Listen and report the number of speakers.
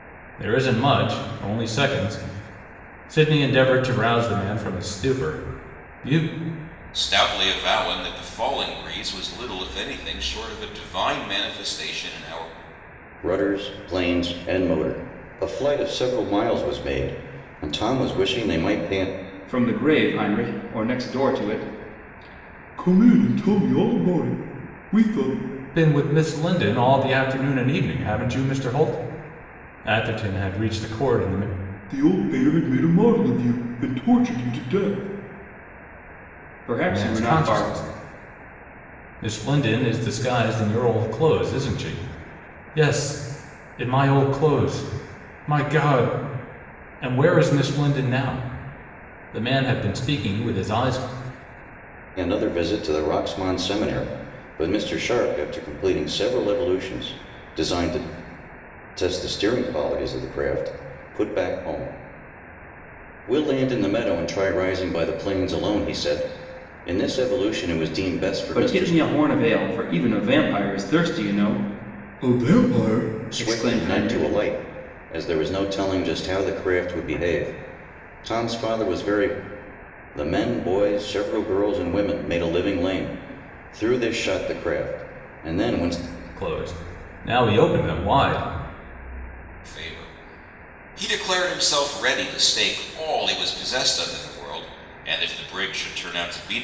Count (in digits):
4